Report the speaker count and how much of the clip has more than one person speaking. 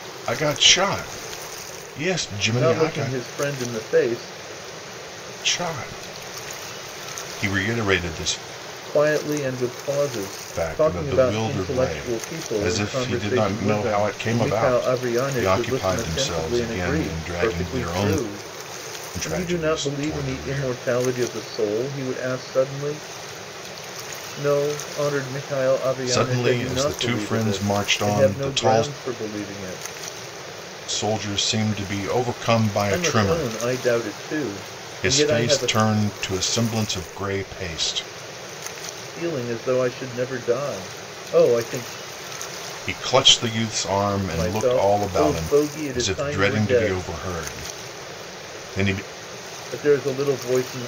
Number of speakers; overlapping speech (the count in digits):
2, about 32%